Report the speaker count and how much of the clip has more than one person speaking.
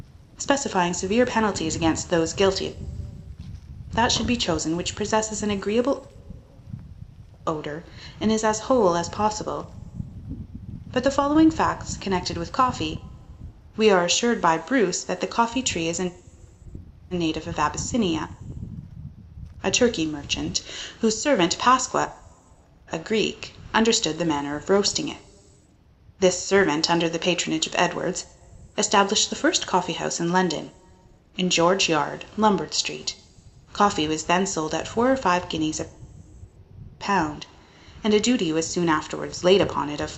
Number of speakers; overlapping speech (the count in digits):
1, no overlap